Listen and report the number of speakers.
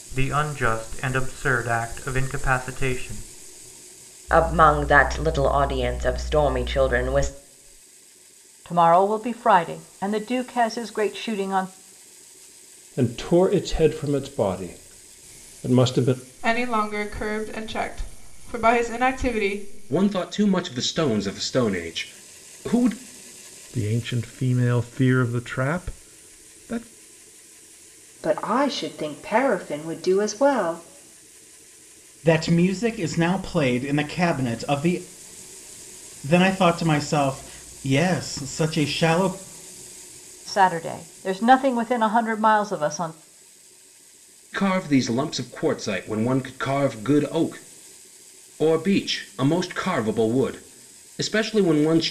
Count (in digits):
9